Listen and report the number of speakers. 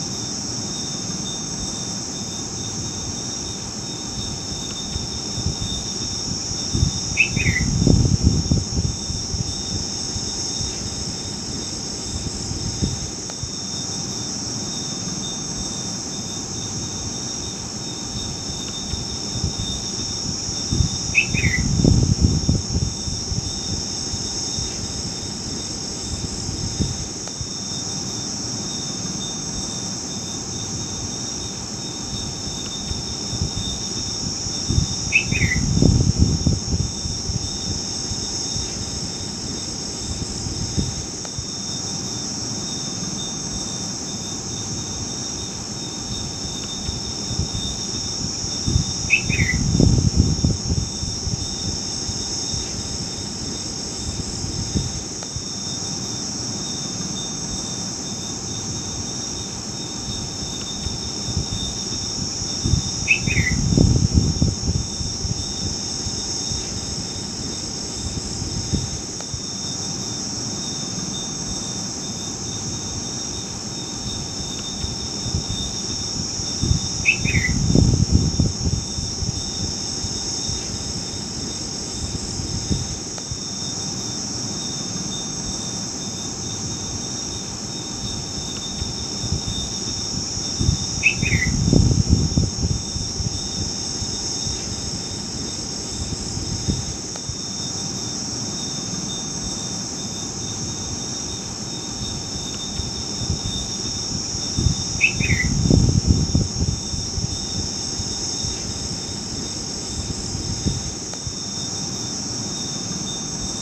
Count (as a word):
zero